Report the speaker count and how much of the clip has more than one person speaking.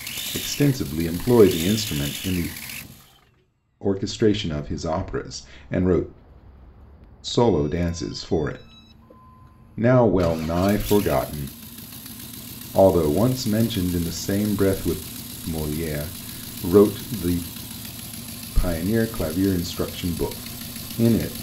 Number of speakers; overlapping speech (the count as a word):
one, no overlap